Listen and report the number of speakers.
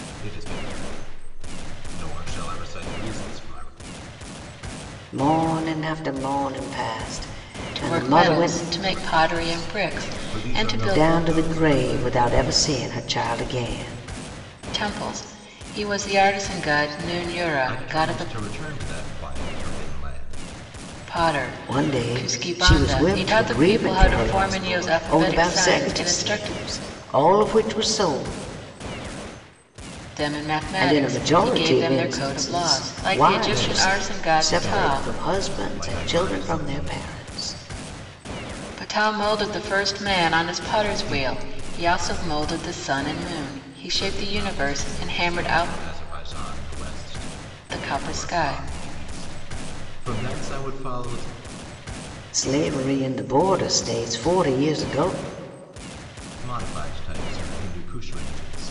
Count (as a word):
three